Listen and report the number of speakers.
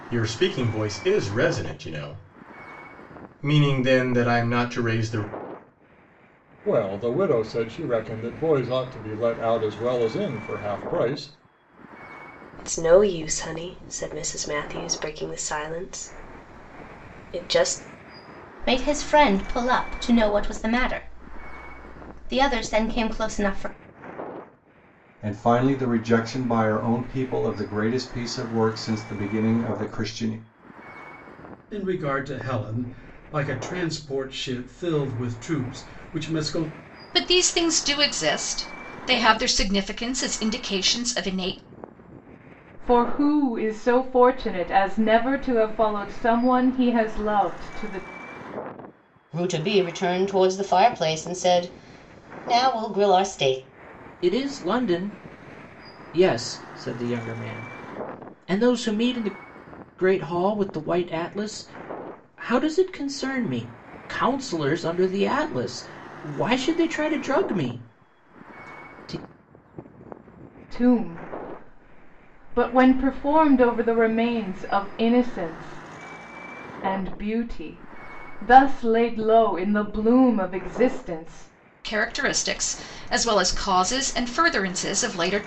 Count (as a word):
ten